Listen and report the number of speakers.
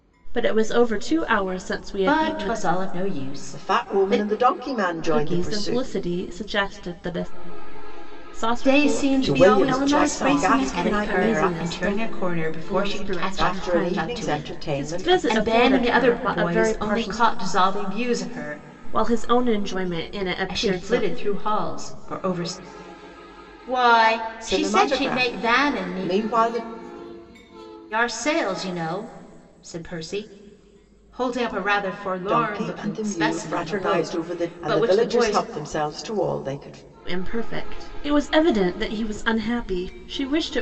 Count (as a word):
three